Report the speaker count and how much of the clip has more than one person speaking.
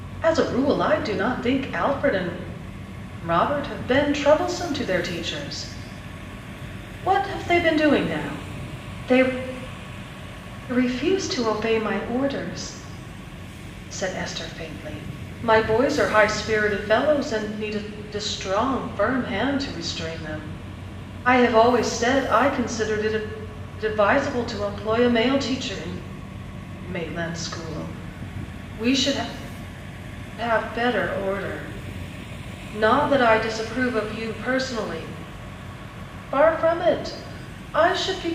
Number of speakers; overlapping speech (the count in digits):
1, no overlap